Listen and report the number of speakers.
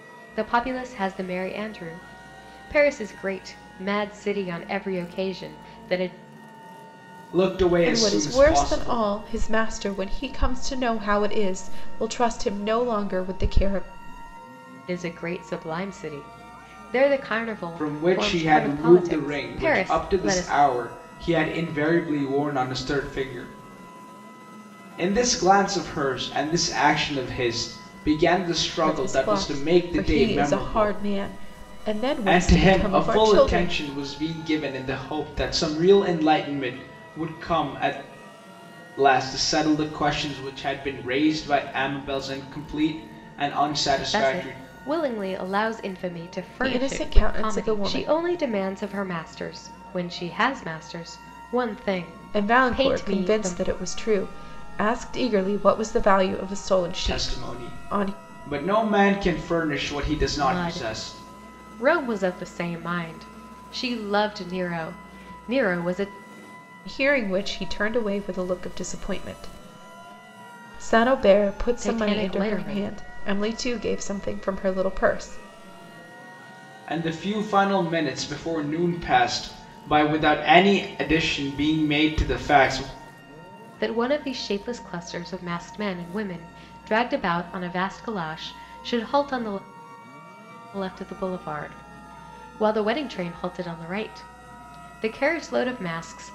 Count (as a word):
three